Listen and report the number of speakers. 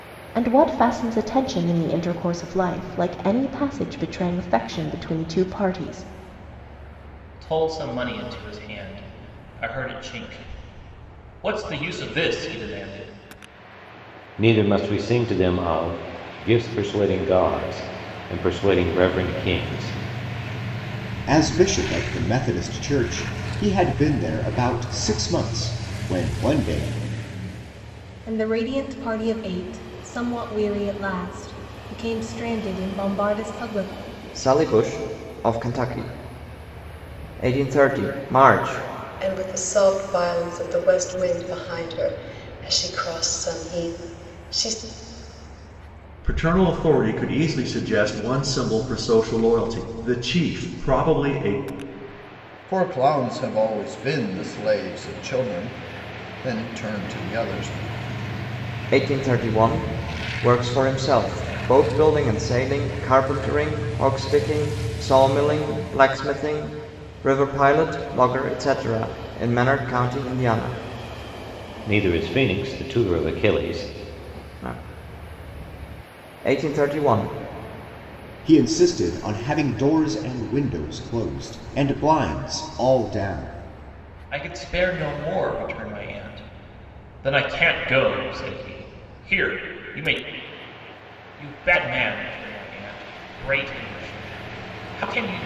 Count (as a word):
nine